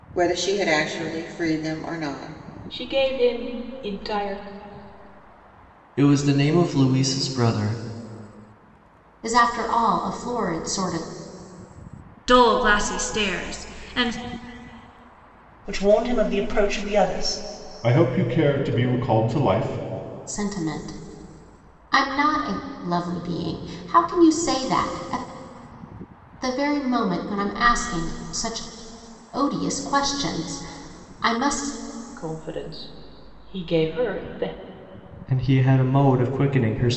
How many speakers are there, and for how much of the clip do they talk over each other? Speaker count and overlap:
7, no overlap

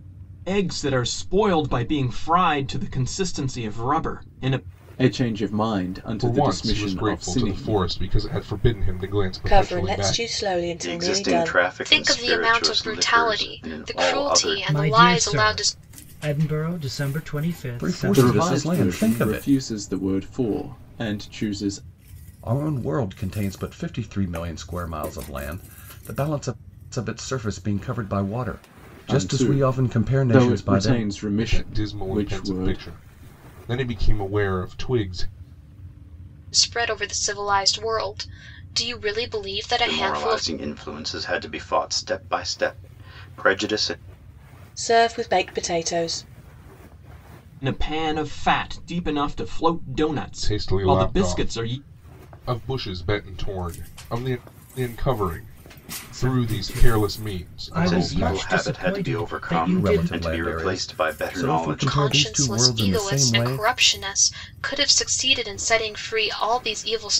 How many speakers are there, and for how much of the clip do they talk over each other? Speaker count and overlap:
8, about 33%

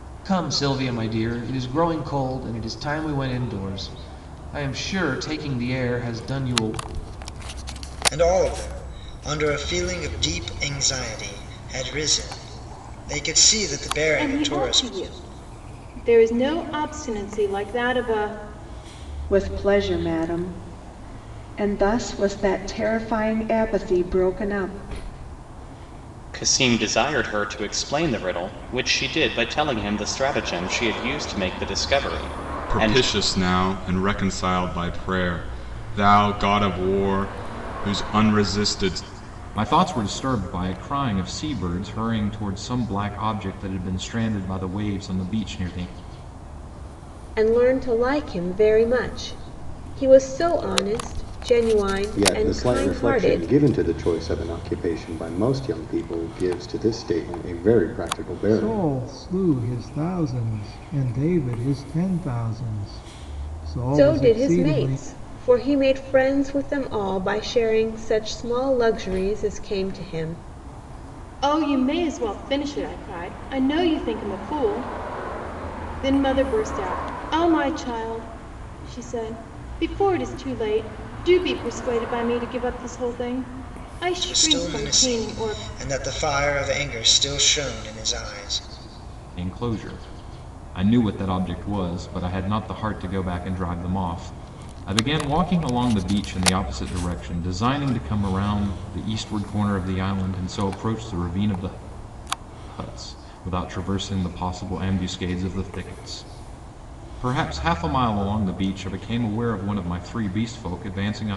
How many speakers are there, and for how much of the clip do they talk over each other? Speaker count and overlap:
10, about 5%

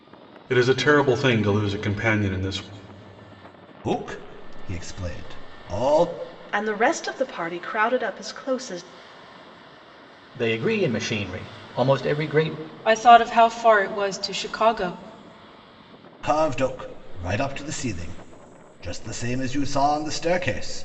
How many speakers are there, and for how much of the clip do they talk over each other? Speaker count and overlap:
5, no overlap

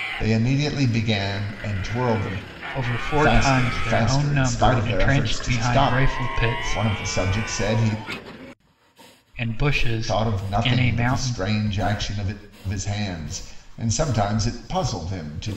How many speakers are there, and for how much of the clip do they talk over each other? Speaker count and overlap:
2, about 33%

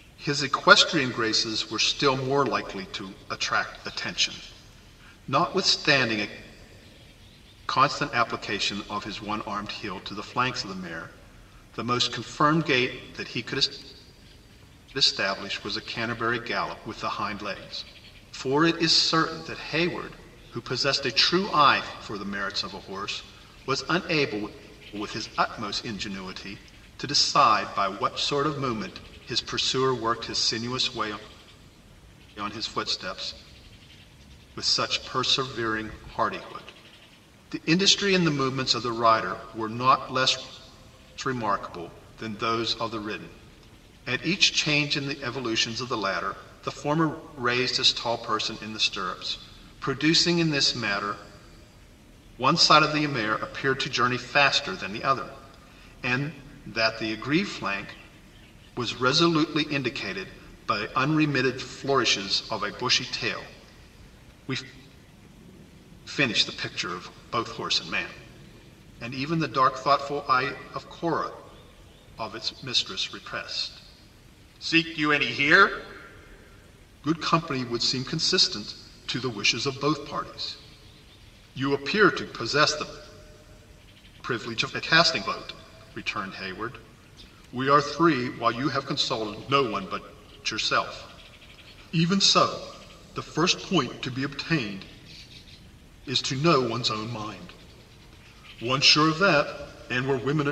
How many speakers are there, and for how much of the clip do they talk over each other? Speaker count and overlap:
1, no overlap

